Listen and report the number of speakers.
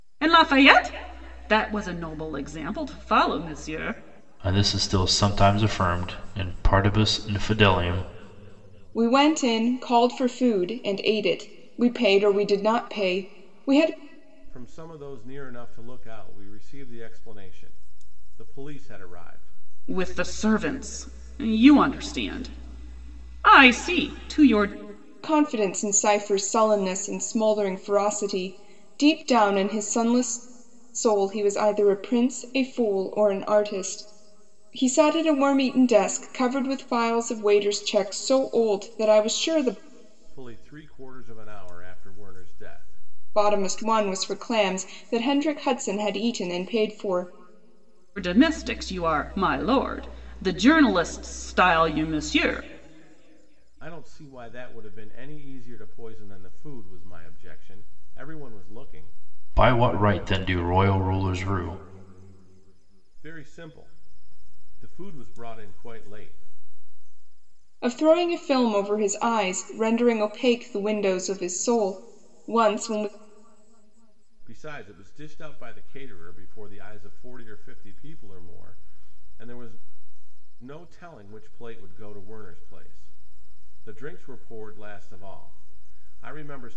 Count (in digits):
4